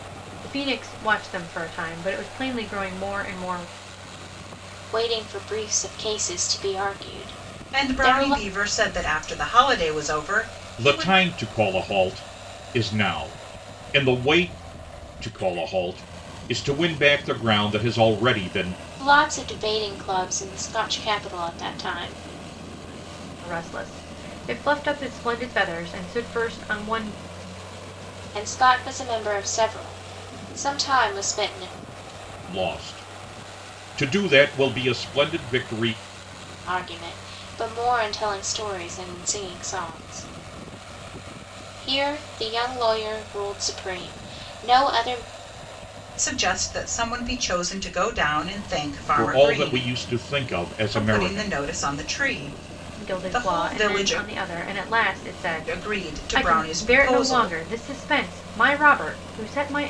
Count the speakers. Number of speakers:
4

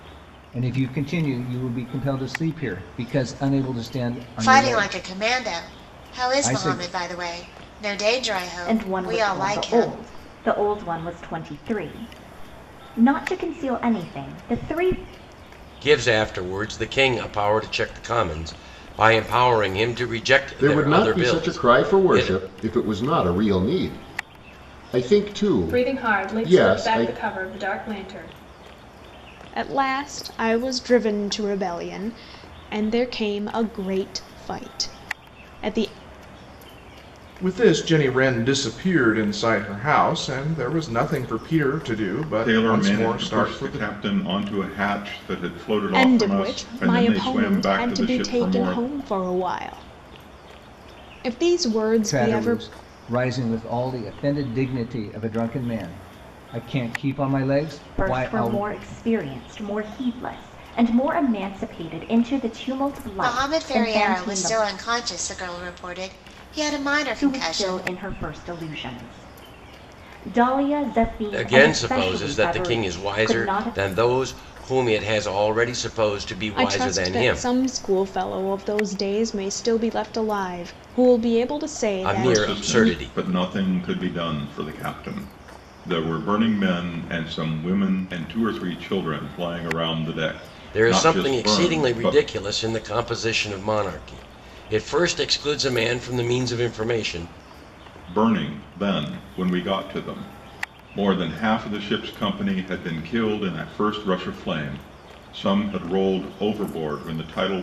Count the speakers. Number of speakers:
9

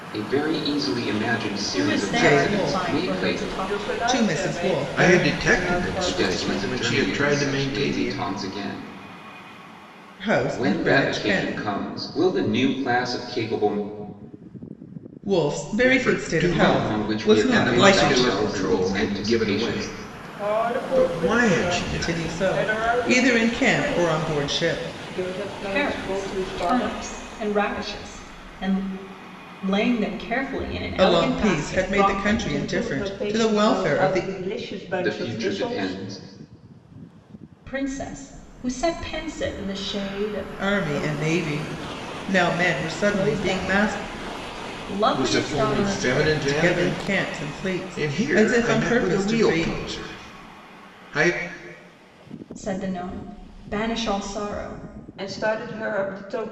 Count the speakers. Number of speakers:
5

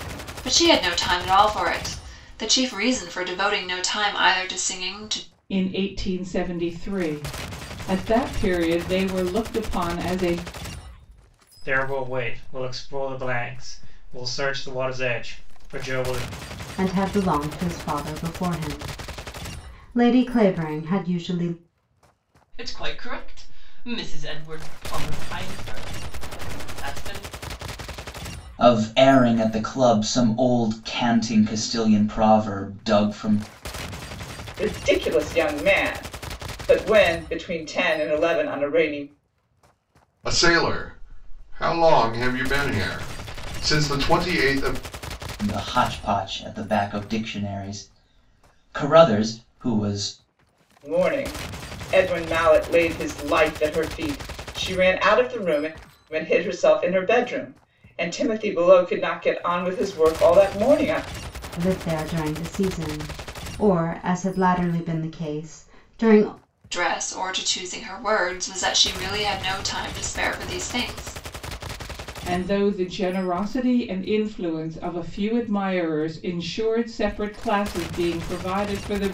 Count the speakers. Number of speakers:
8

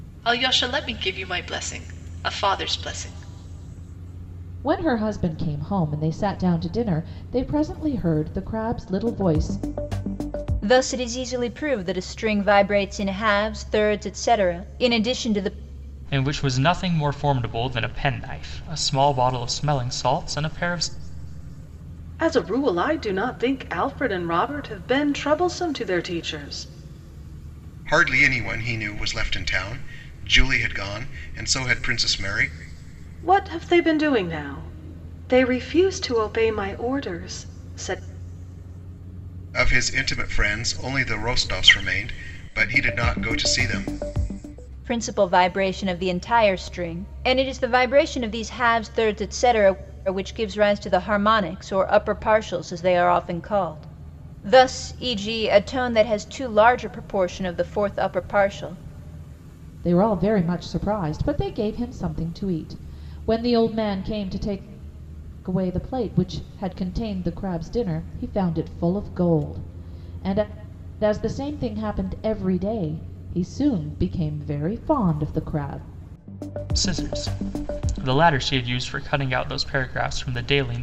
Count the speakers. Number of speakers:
6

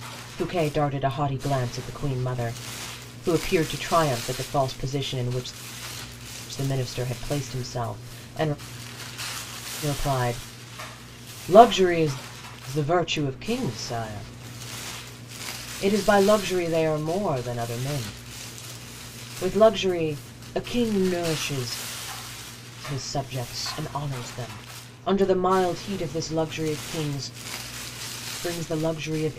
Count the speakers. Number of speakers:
1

